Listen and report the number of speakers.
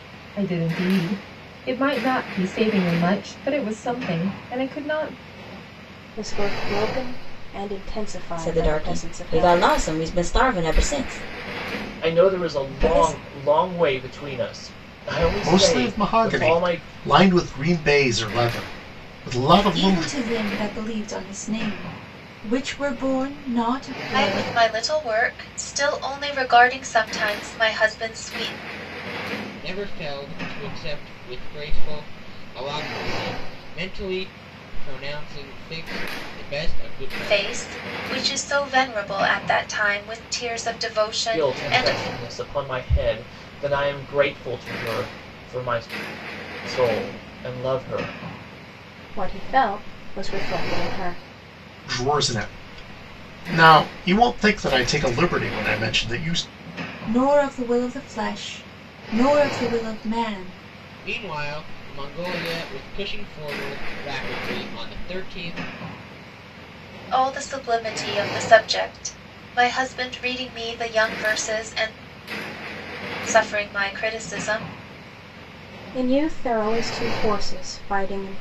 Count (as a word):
eight